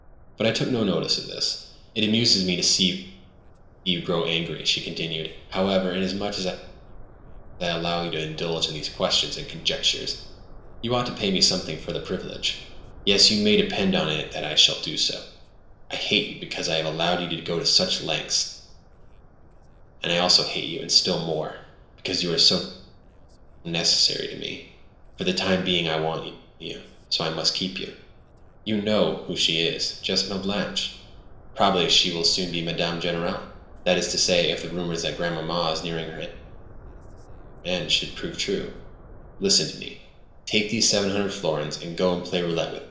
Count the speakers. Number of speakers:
one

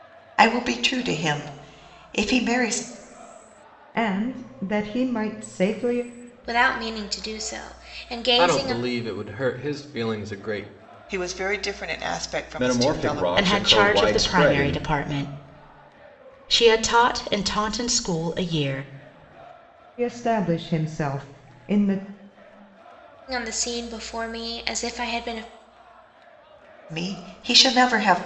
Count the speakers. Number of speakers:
seven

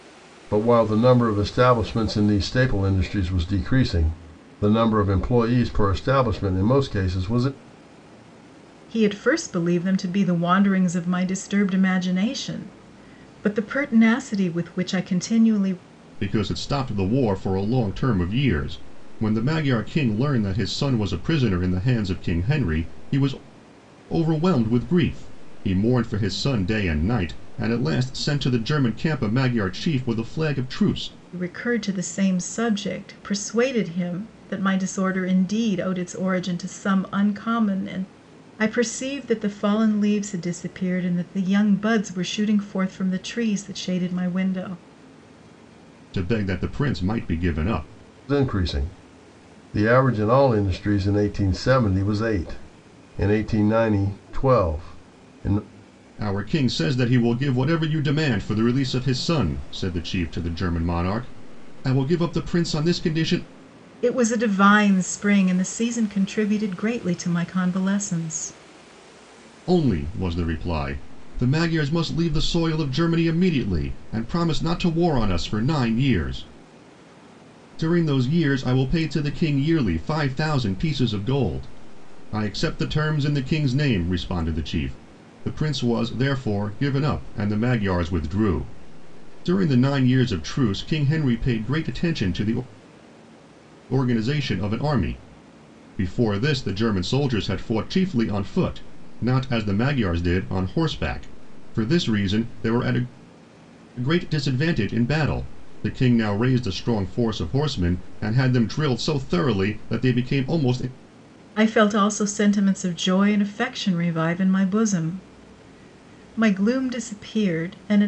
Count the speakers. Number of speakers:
three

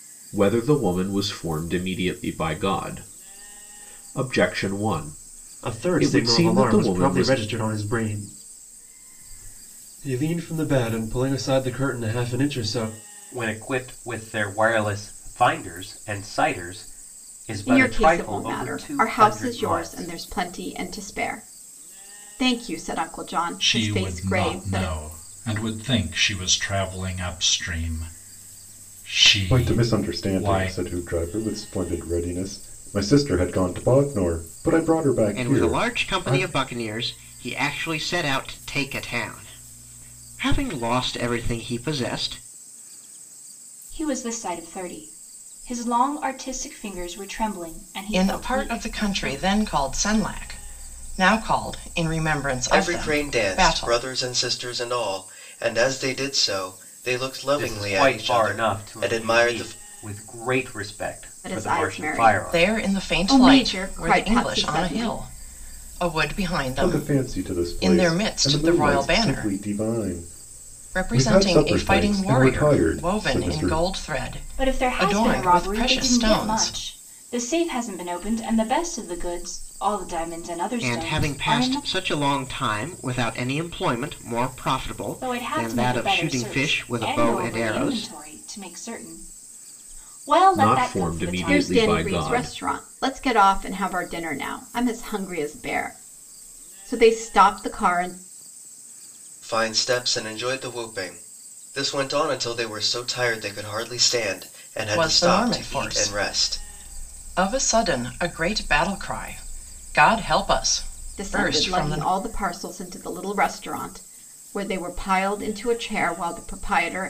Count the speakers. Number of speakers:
ten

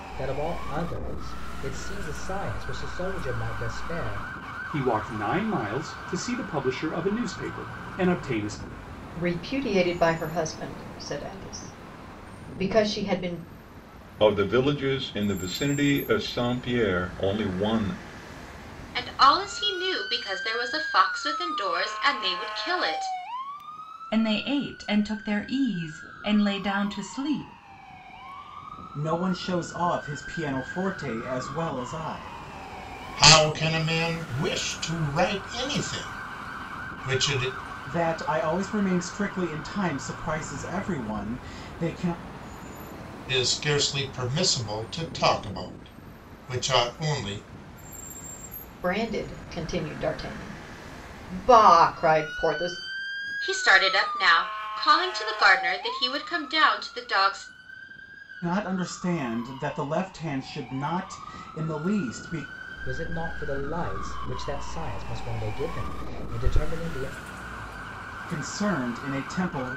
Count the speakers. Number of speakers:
eight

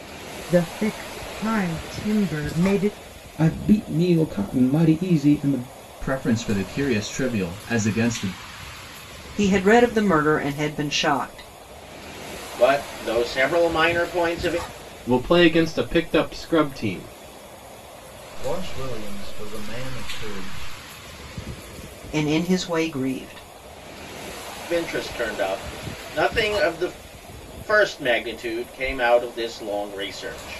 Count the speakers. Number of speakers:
seven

